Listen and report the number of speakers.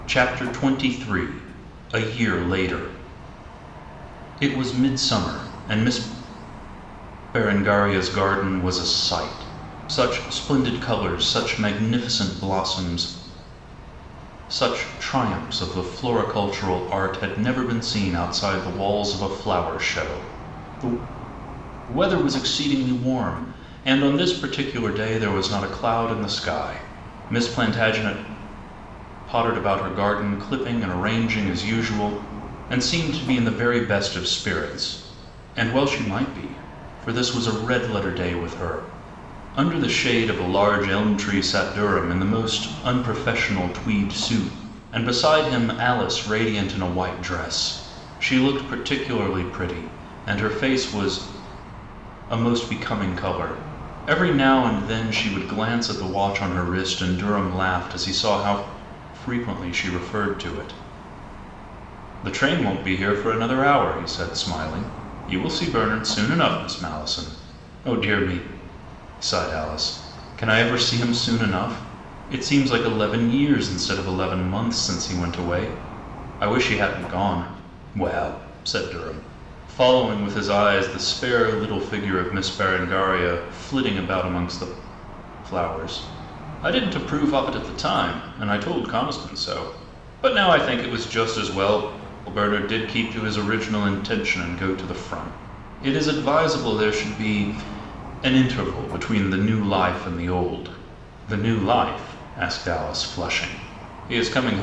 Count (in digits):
1